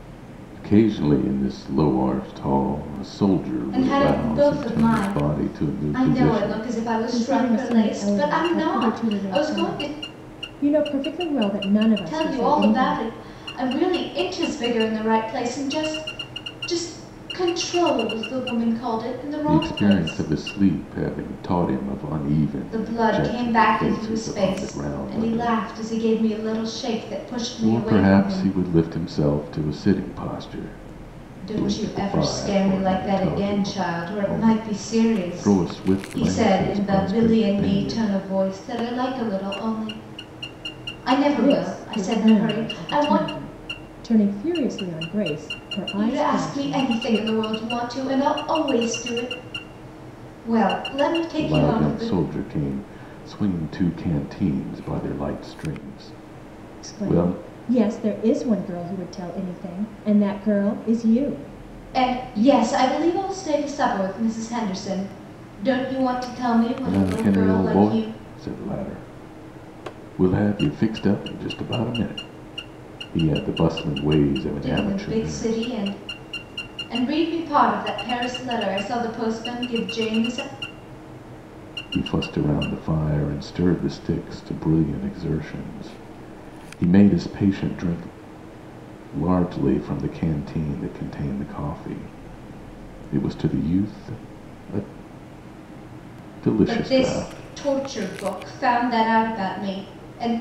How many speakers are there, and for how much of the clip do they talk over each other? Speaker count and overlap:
3, about 27%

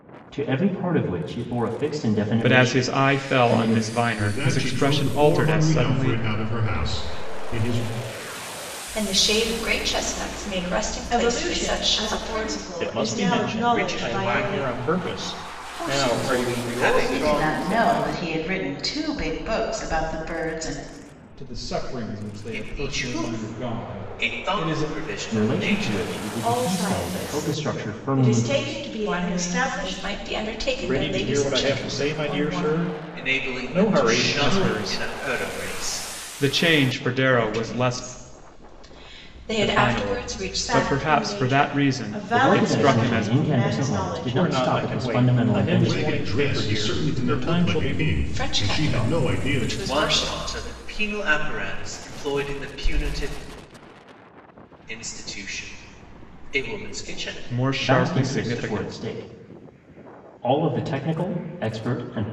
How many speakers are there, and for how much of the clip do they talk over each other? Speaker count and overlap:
10, about 56%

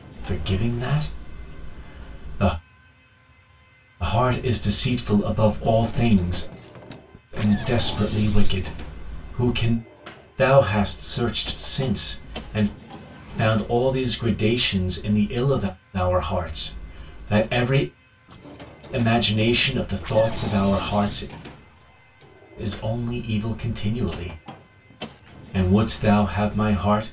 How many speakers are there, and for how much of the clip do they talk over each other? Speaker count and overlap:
1, no overlap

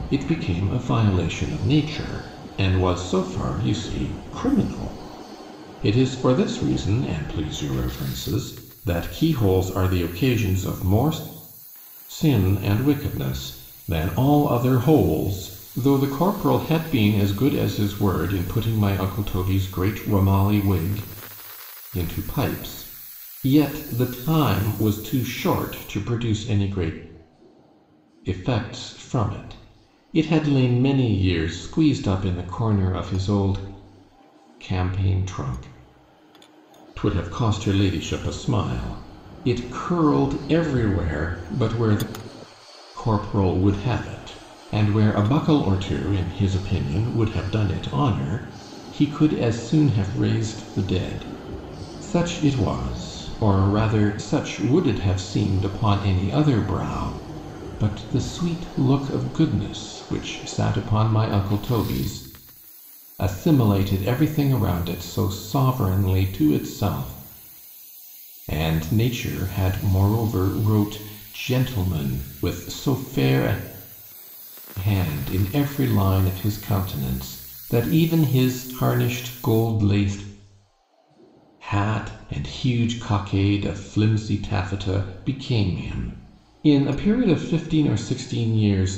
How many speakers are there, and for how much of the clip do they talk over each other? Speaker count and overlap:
1, no overlap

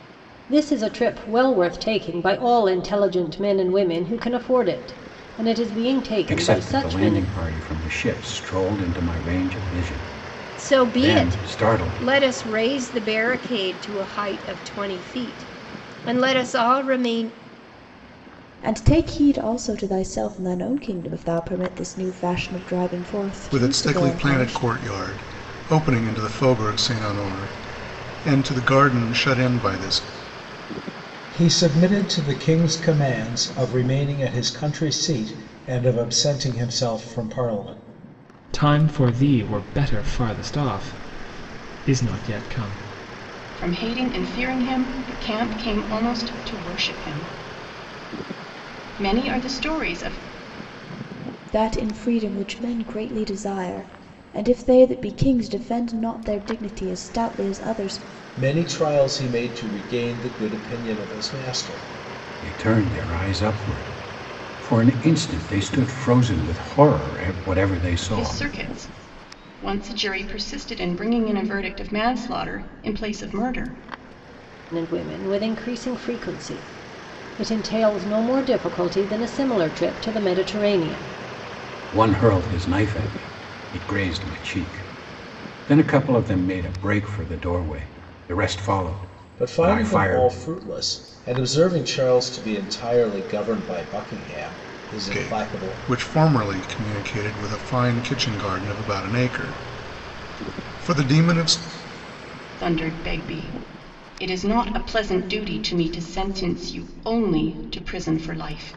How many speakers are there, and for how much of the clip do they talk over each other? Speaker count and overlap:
8, about 5%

